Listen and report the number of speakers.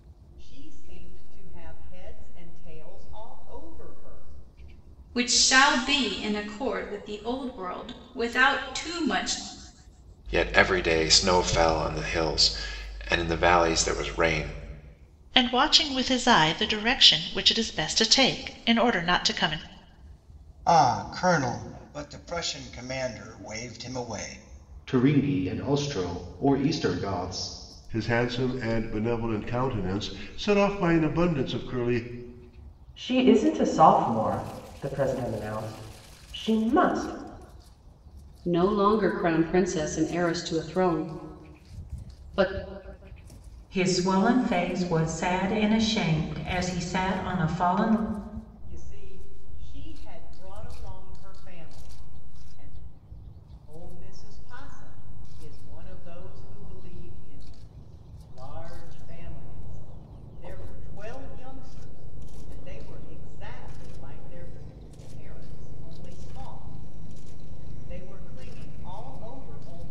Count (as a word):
ten